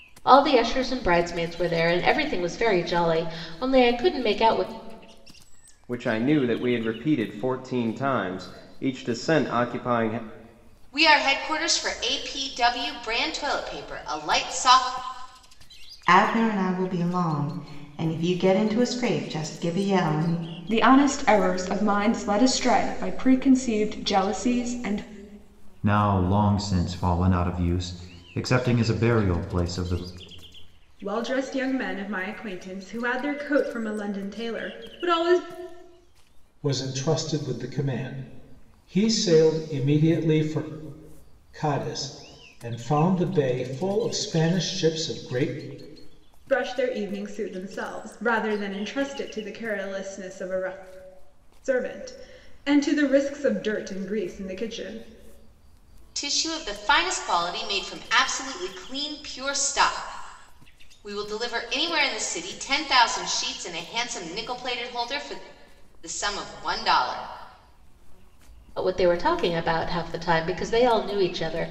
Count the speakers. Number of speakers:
eight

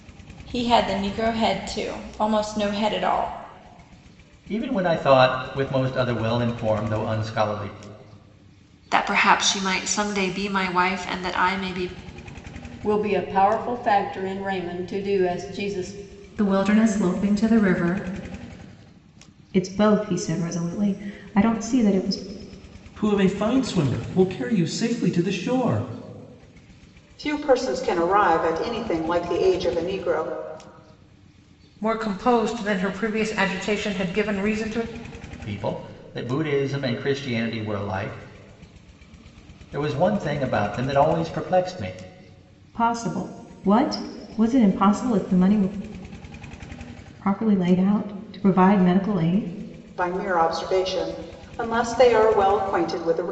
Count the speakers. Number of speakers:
nine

